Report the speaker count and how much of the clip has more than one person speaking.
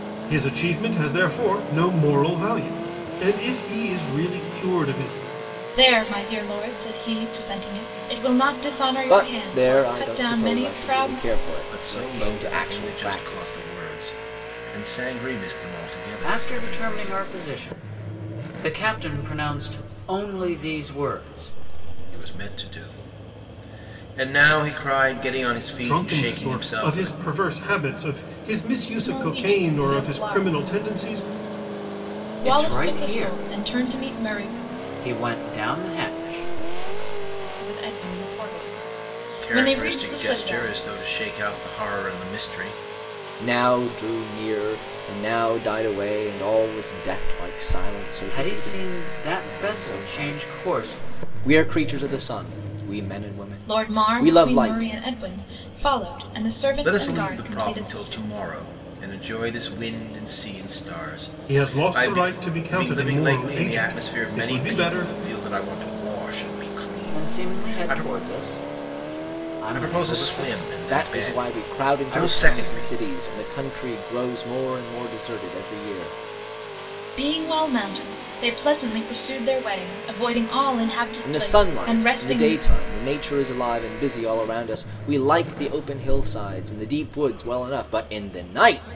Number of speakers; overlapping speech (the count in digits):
5, about 30%